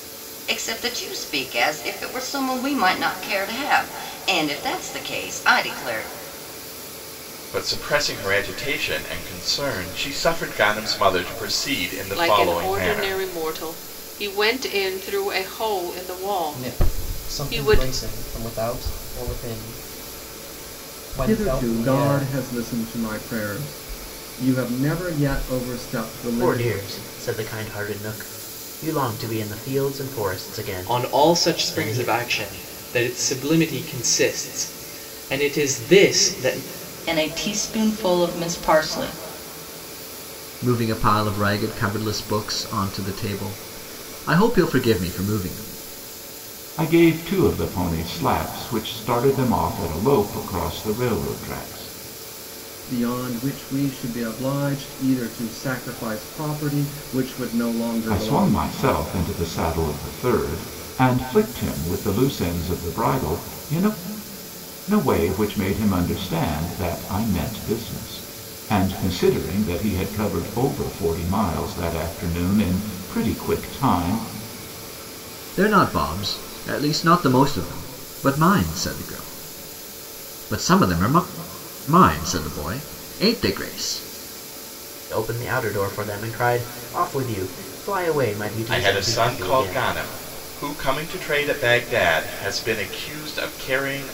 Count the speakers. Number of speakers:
ten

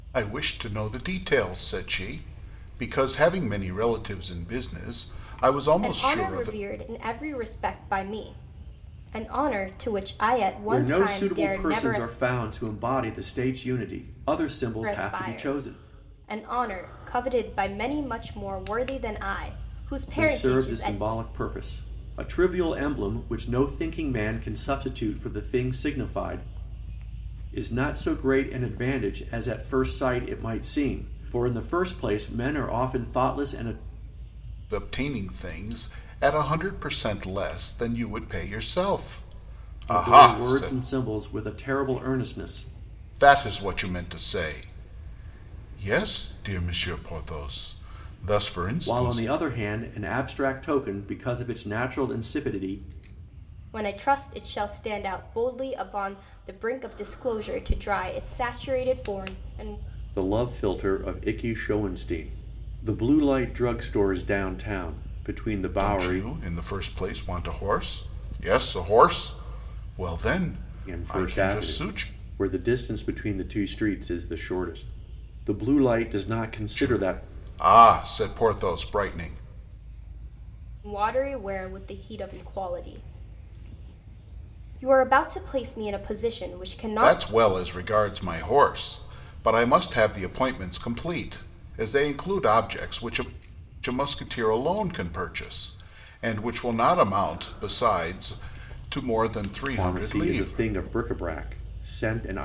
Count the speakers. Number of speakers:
three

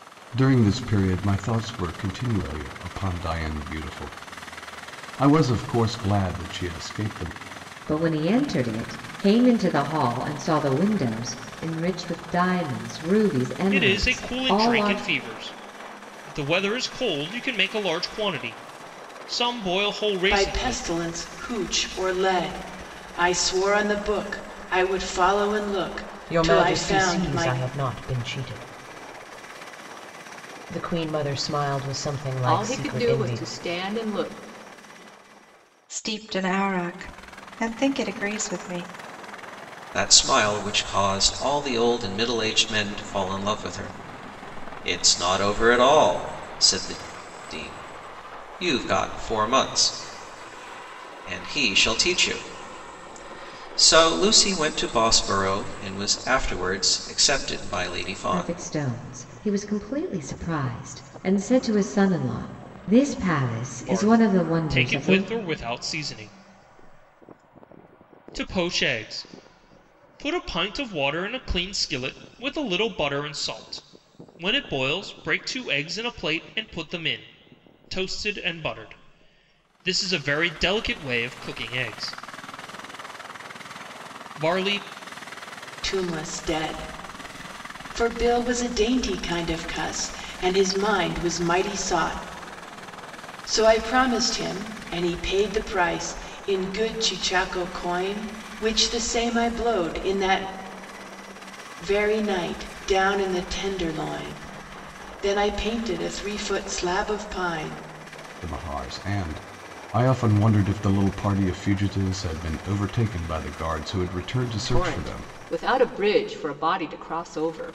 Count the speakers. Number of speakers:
eight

